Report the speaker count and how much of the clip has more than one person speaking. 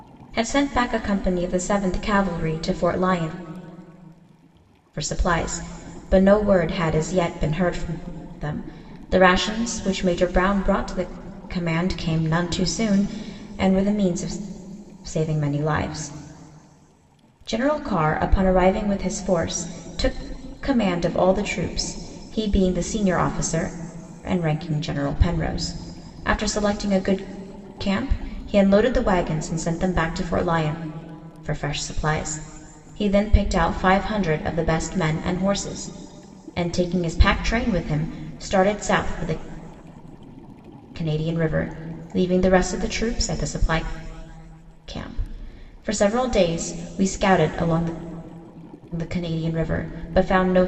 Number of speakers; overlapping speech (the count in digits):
1, no overlap